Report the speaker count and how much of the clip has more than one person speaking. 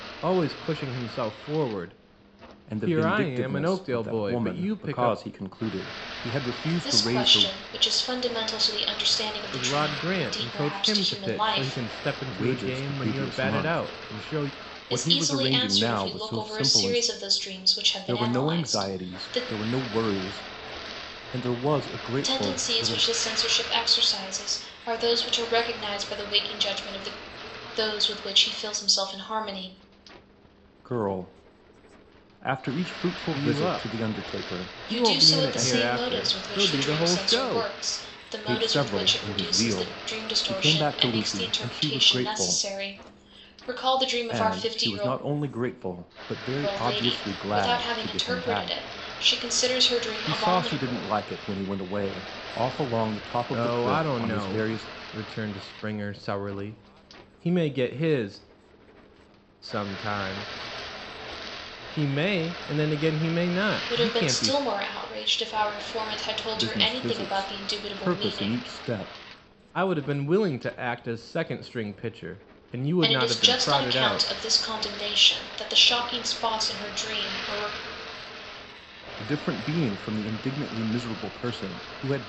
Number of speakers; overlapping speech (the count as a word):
three, about 37%